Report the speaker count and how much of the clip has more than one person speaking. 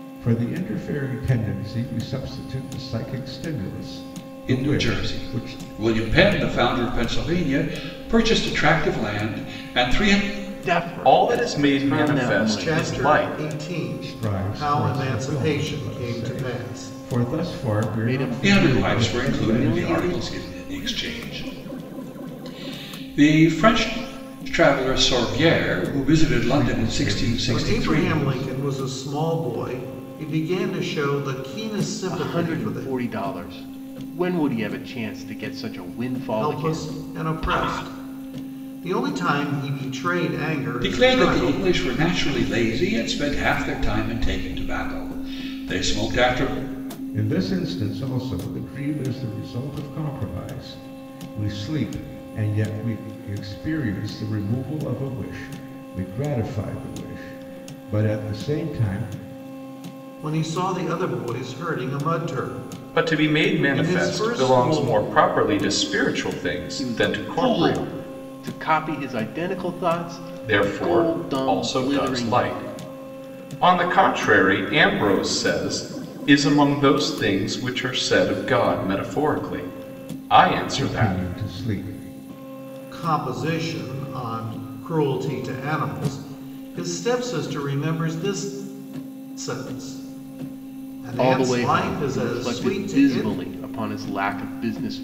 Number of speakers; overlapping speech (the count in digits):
5, about 23%